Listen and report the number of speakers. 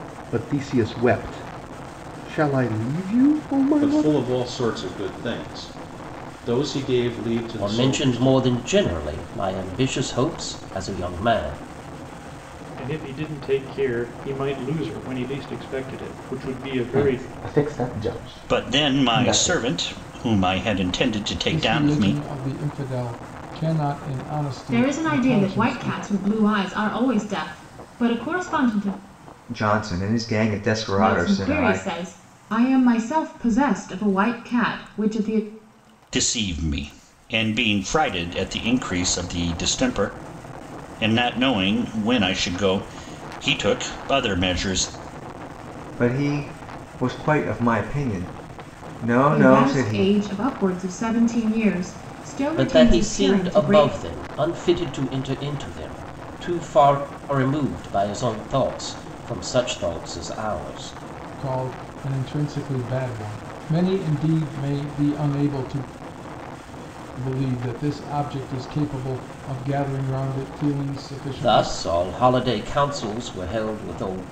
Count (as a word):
nine